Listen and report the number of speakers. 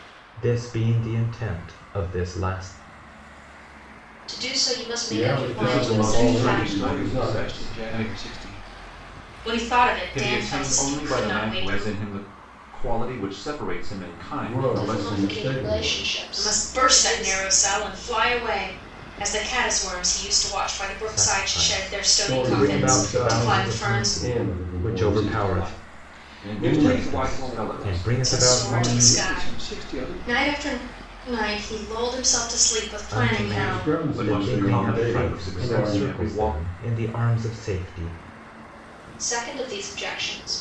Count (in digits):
6